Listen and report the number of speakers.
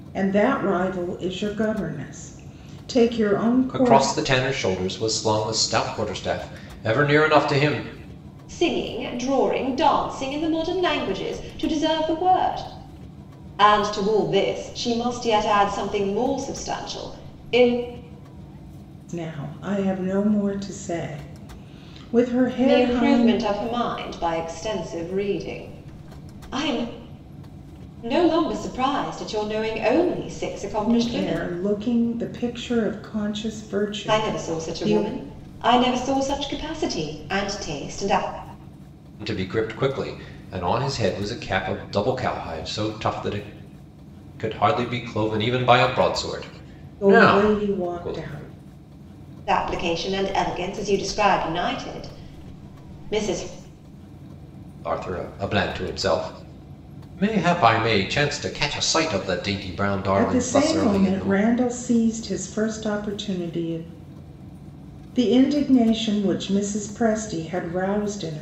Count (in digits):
3